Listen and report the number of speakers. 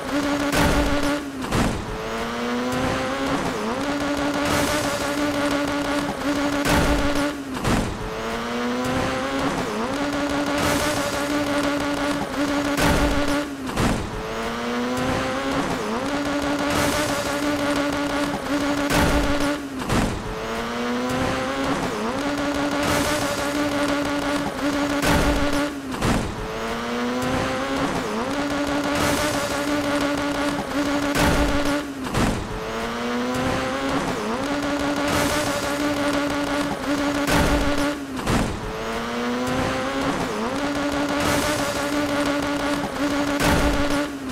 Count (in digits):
0